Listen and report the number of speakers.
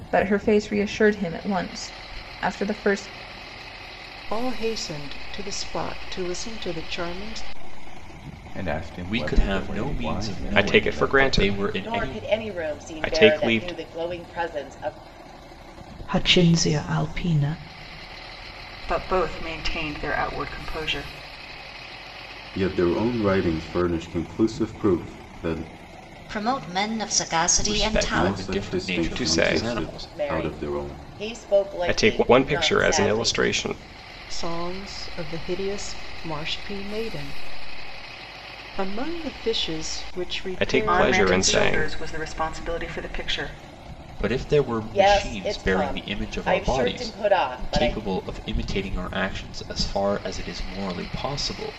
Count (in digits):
10